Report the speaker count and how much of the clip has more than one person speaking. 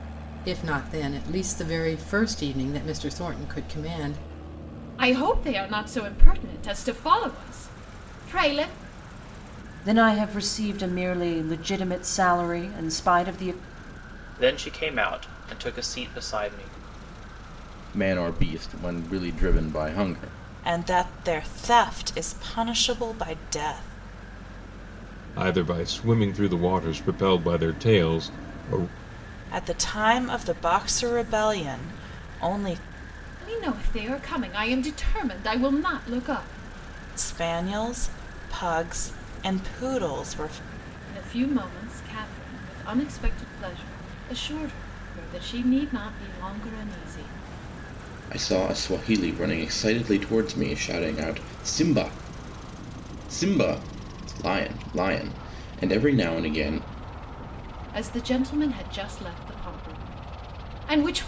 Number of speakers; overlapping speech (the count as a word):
seven, no overlap